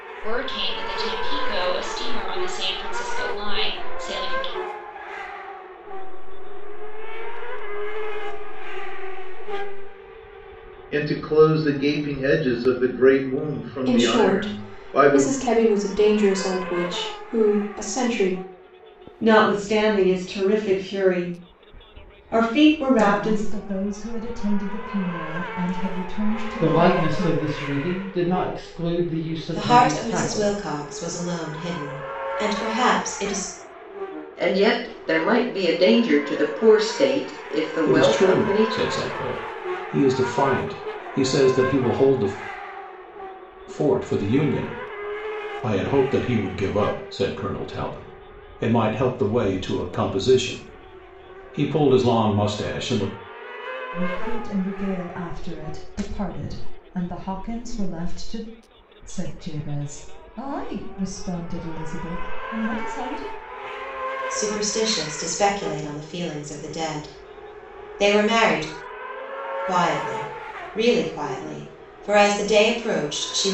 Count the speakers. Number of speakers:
10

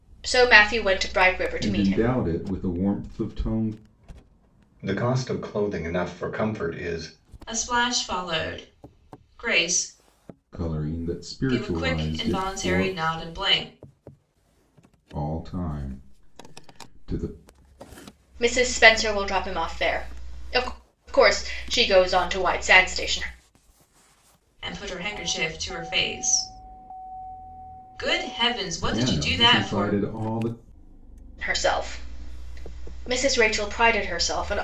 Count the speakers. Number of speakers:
4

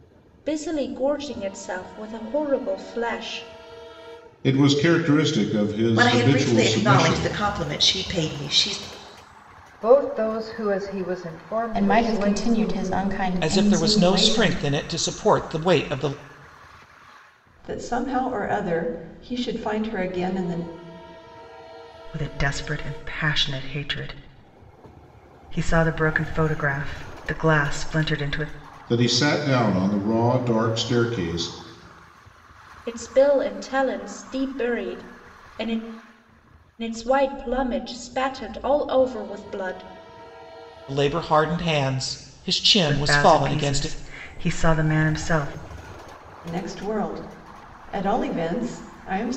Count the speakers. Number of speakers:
8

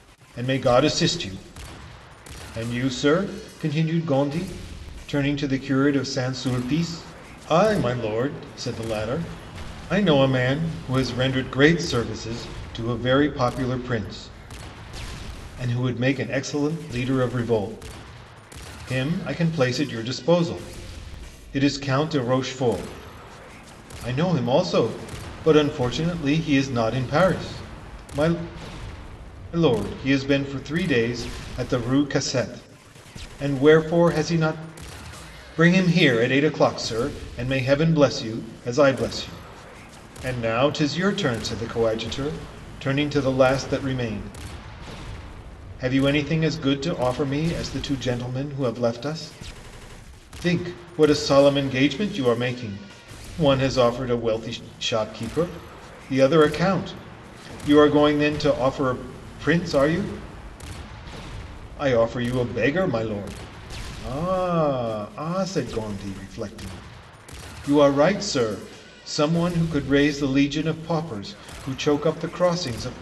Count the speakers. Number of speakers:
1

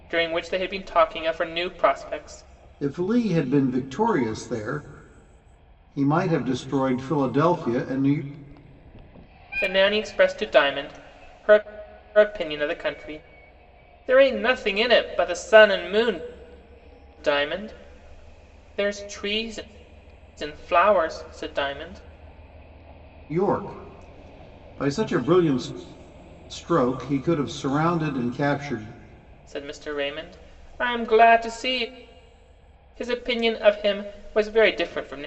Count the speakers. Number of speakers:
2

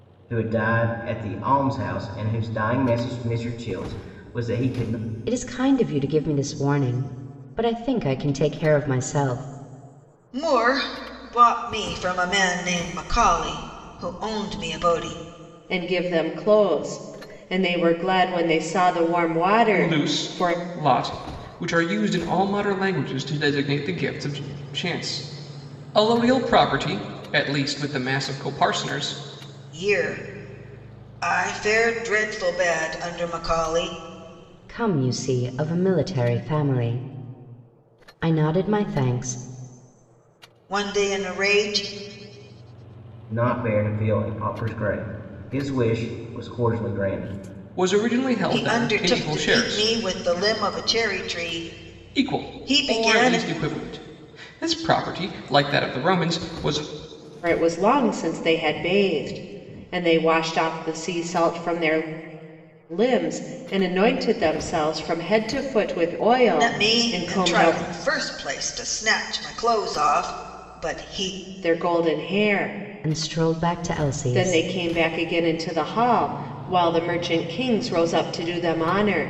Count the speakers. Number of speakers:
5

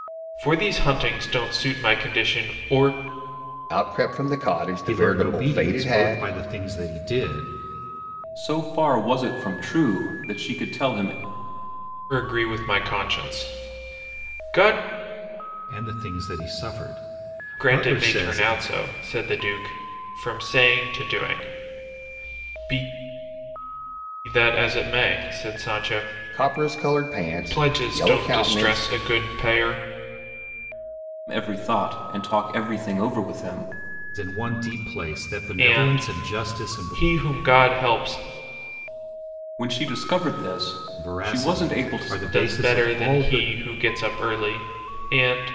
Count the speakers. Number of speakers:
4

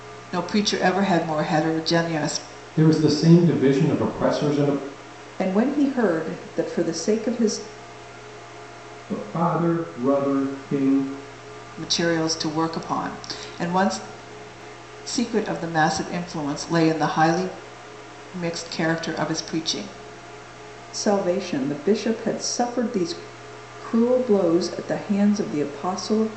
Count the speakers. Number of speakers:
4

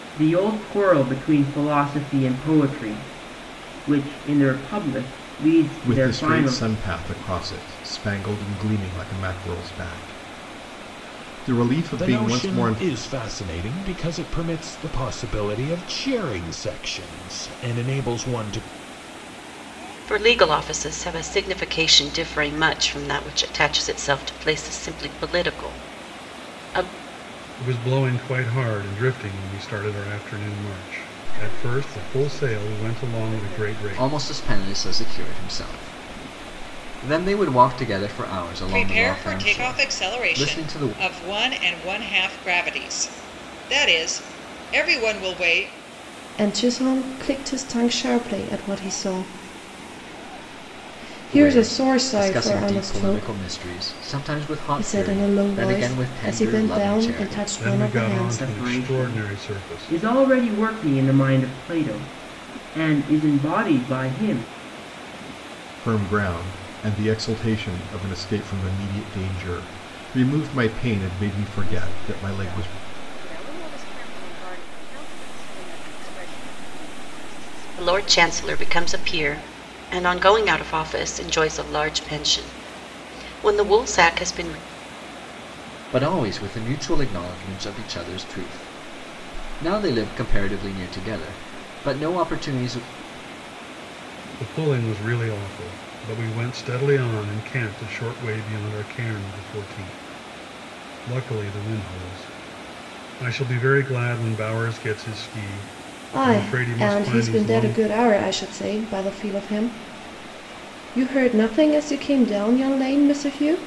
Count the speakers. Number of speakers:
9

